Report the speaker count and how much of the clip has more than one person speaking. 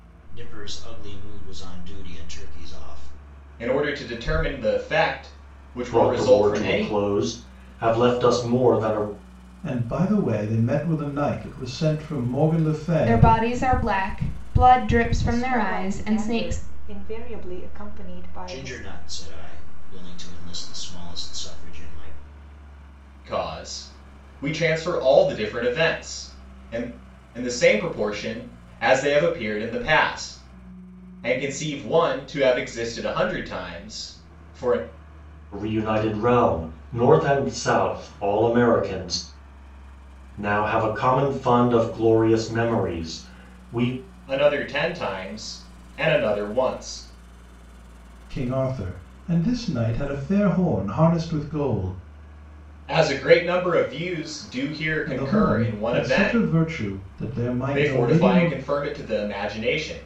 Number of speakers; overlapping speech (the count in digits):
6, about 10%